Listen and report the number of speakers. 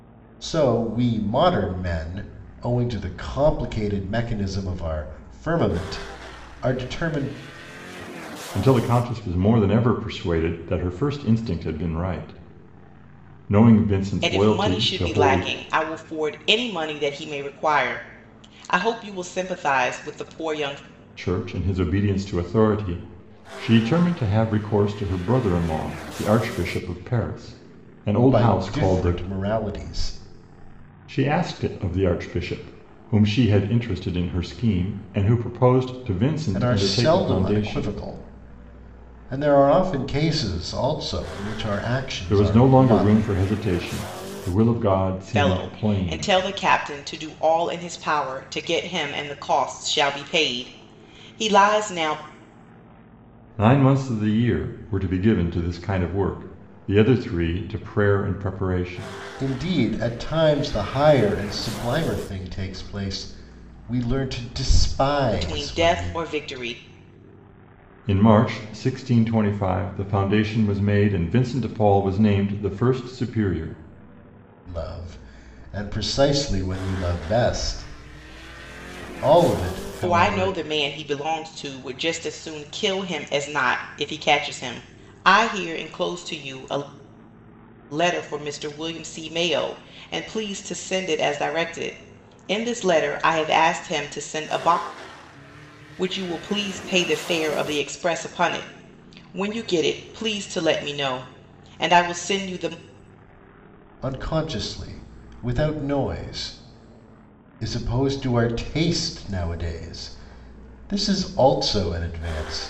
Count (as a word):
three